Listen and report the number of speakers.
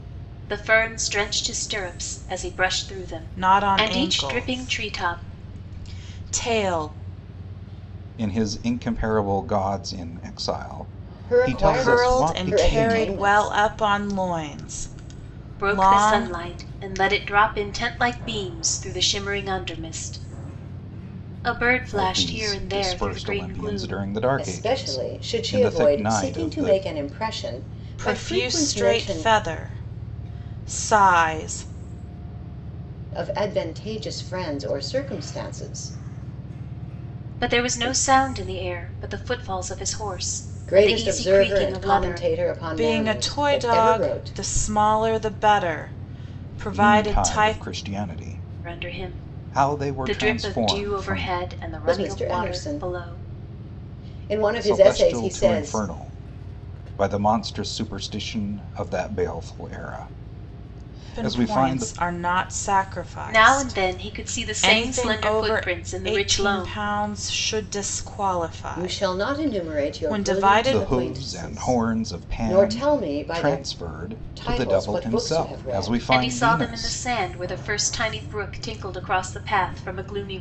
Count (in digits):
4